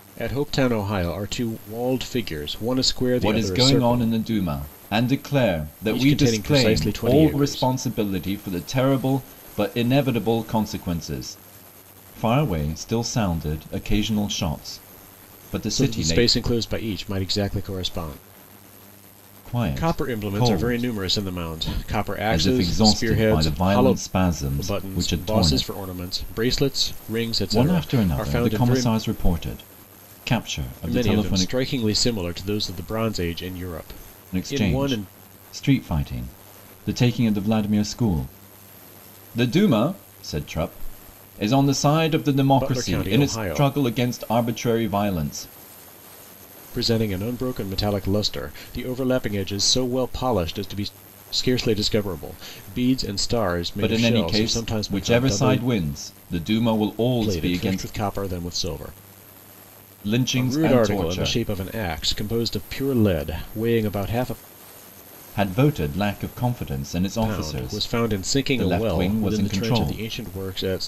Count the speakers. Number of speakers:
2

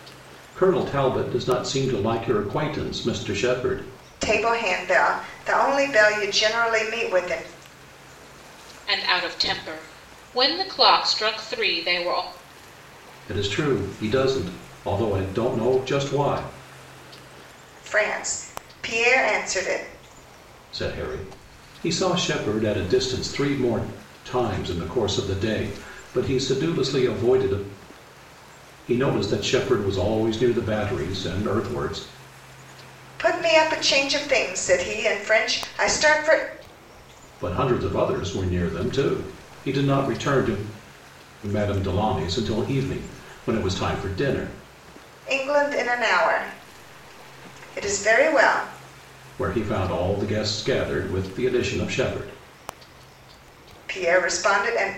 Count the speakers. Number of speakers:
3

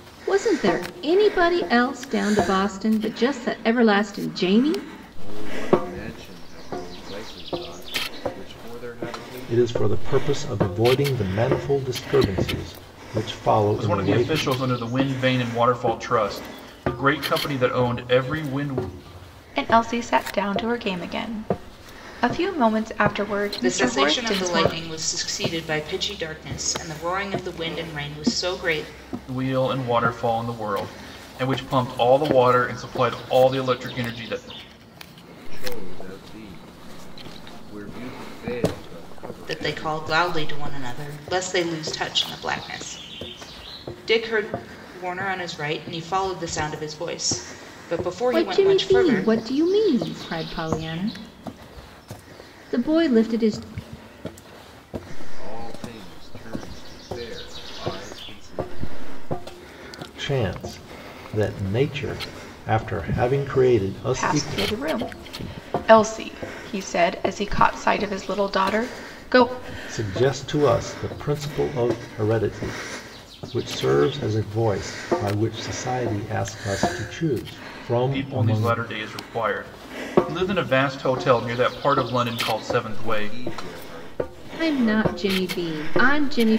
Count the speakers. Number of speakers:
6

